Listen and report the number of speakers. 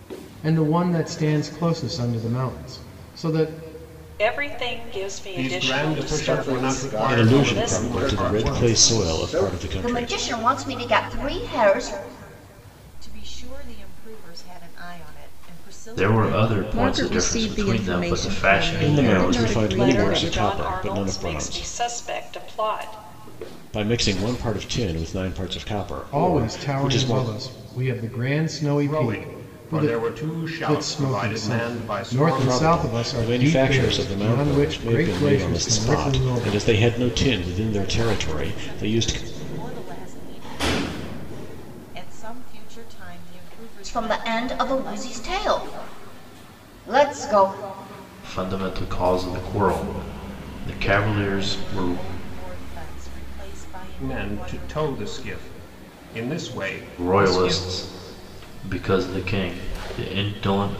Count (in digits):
9